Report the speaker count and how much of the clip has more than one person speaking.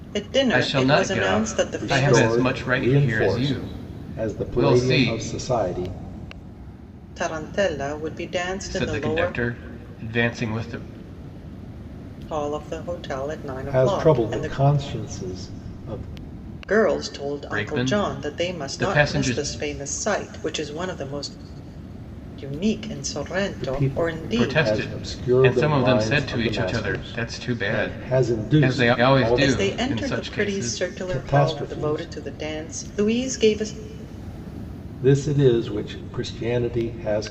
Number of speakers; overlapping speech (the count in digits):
3, about 44%